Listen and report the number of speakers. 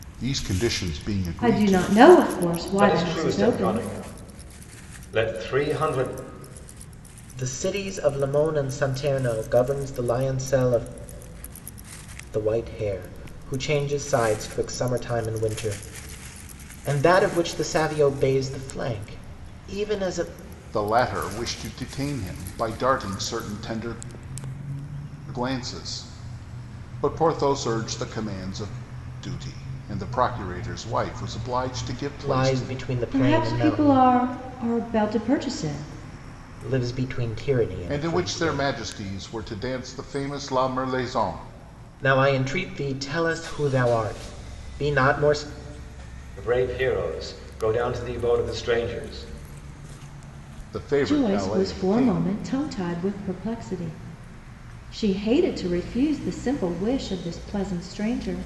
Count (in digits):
4